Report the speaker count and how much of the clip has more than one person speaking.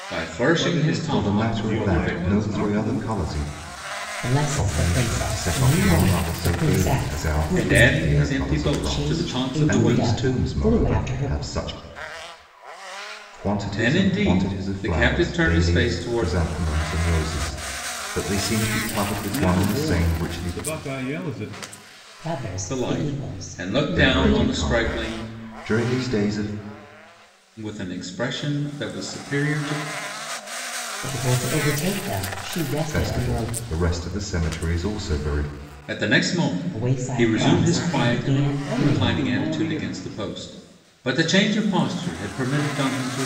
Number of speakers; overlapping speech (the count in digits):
4, about 46%